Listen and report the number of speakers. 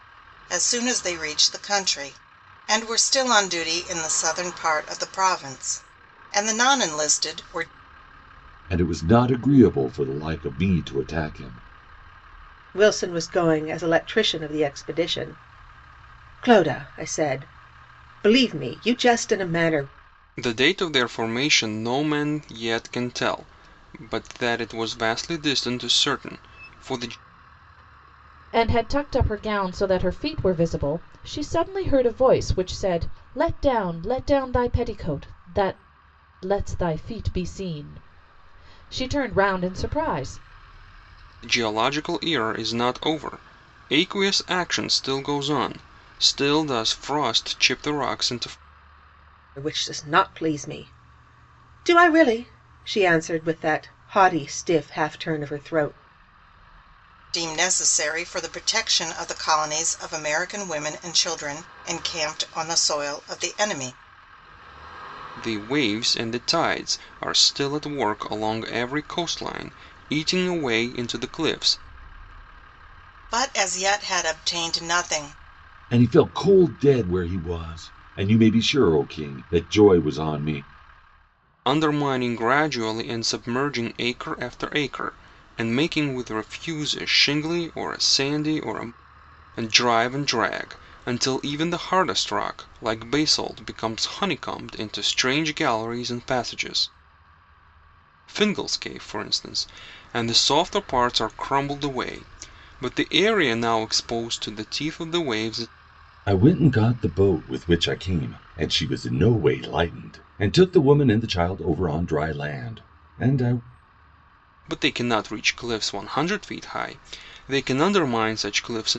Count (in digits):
5